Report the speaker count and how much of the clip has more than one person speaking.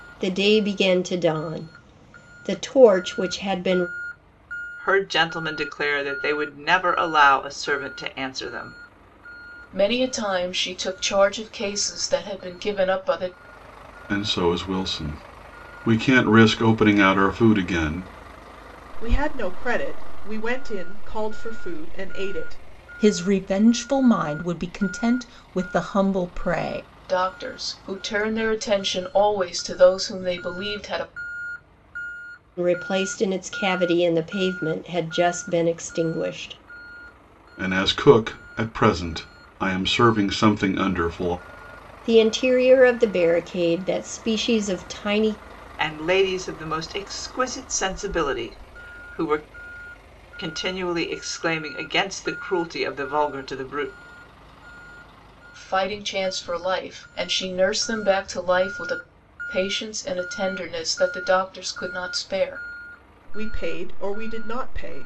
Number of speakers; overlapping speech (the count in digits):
6, no overlap